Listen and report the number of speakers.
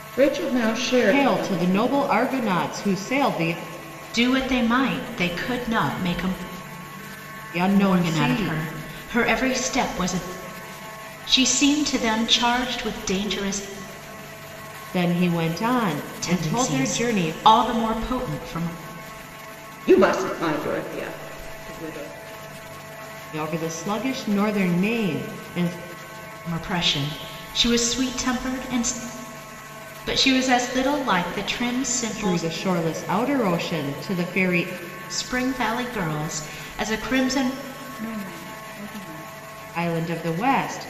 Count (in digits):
3